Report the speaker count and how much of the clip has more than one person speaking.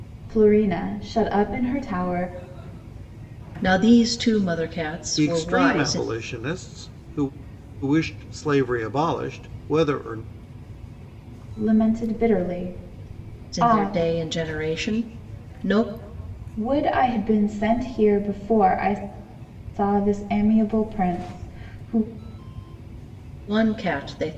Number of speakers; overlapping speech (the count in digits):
3, about 6%